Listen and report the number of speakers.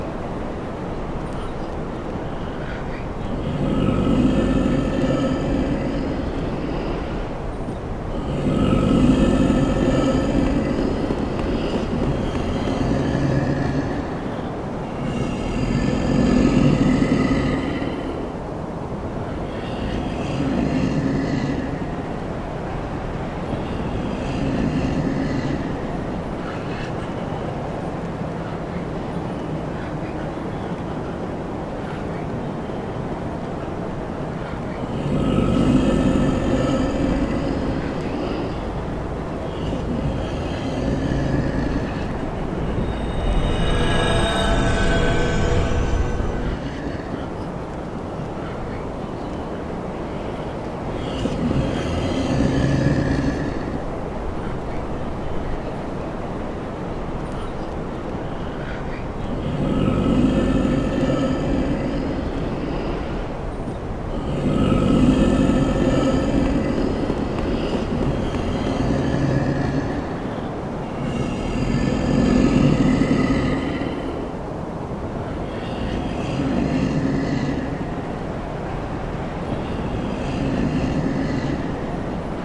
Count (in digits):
0